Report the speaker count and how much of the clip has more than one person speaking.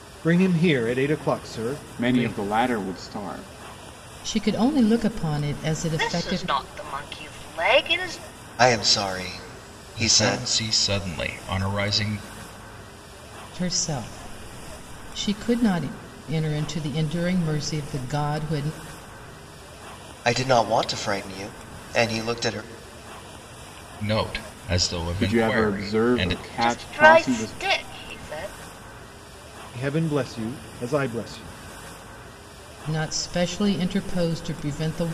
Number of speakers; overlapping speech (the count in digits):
6, about 11%